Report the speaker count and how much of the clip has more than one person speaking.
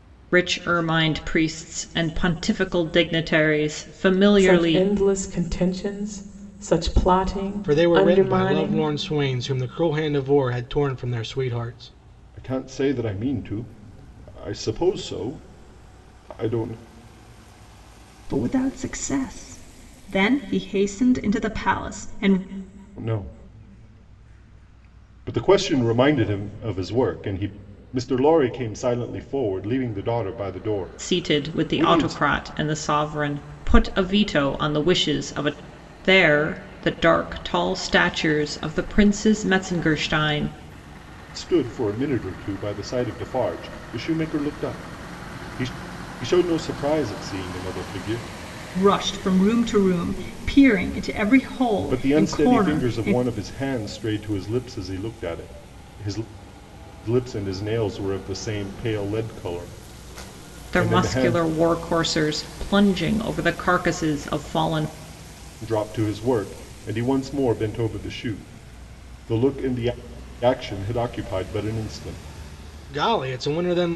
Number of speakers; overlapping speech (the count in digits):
5, about 7%